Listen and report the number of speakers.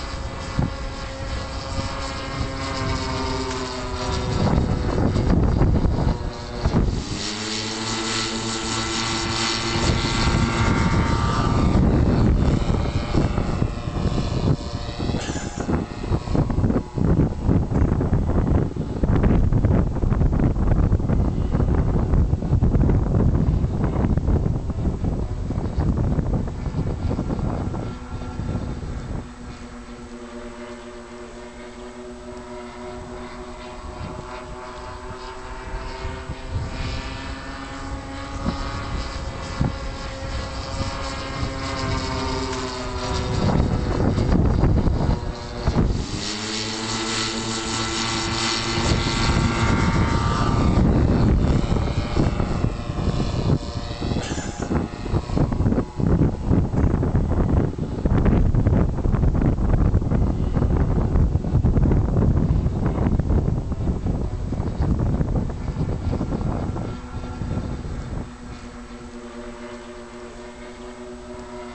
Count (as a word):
zero